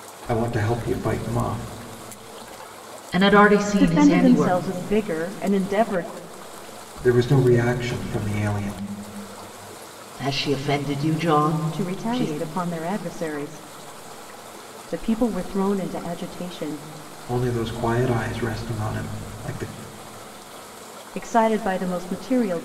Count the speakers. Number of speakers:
3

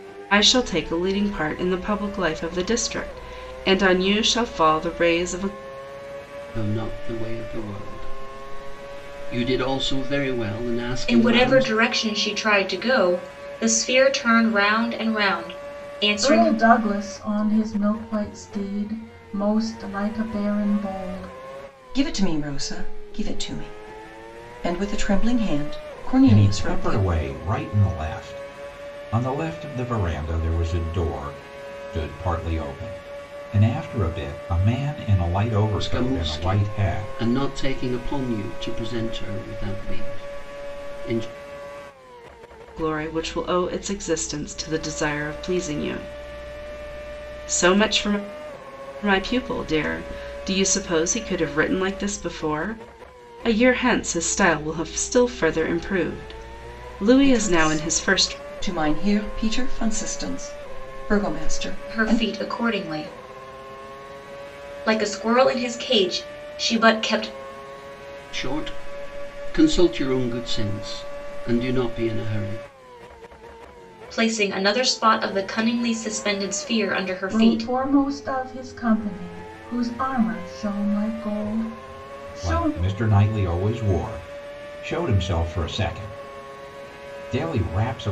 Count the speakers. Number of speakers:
6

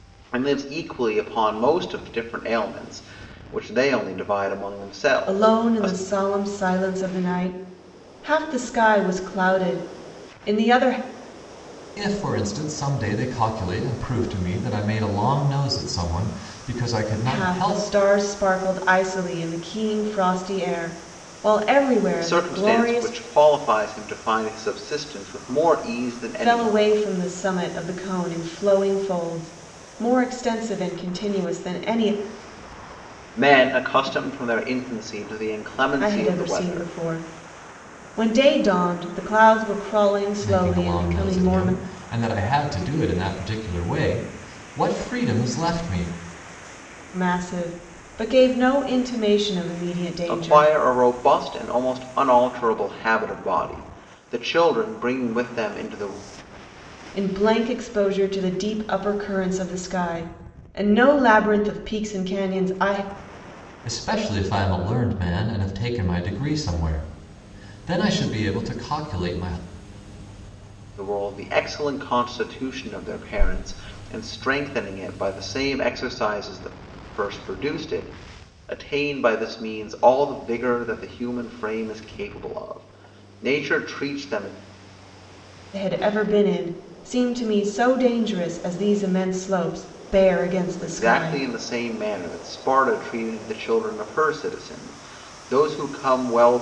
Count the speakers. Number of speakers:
3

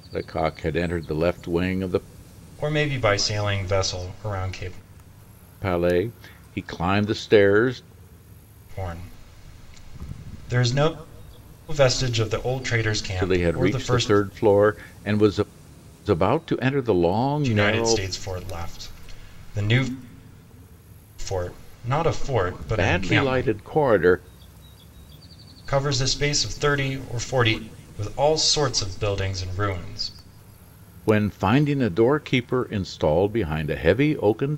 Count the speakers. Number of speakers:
2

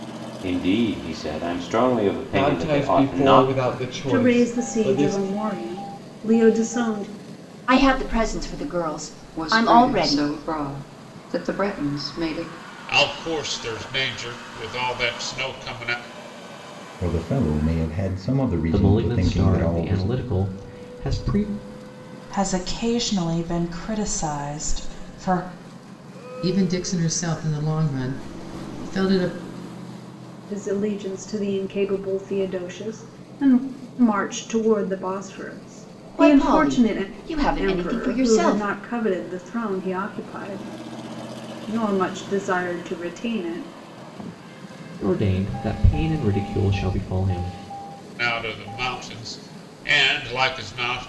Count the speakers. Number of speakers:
10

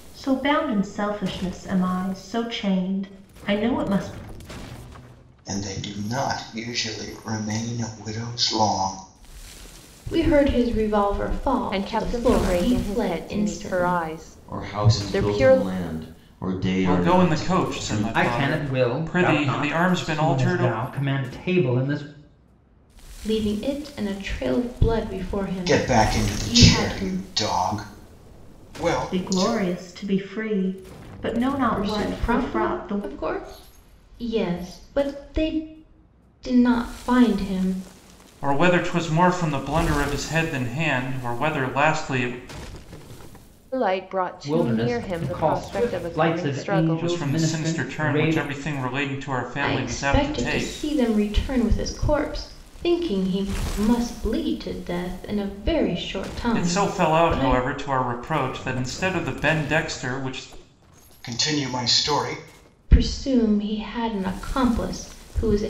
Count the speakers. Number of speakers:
7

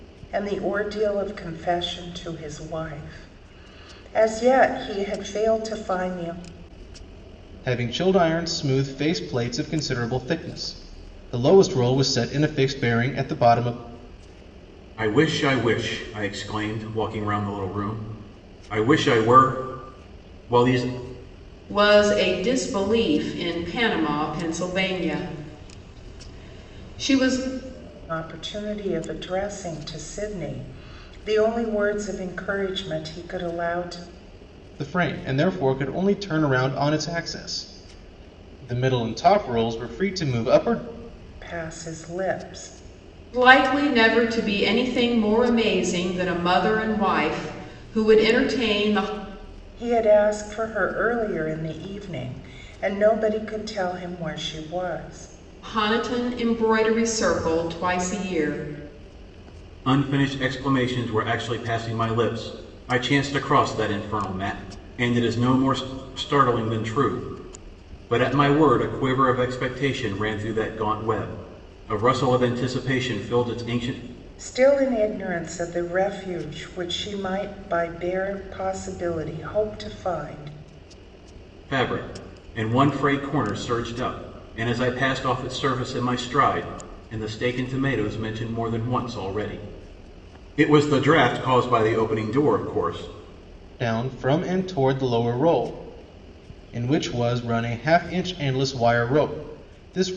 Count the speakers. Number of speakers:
4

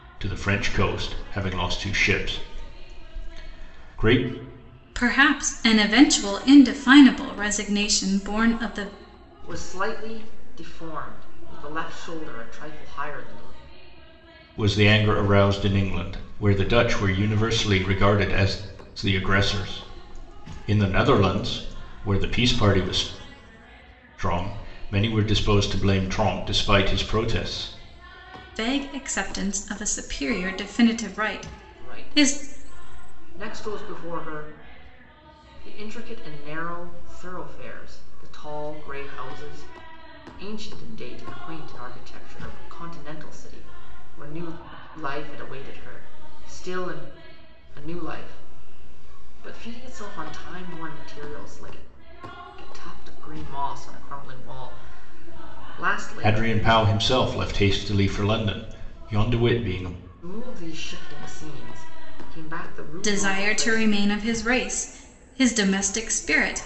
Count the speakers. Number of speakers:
3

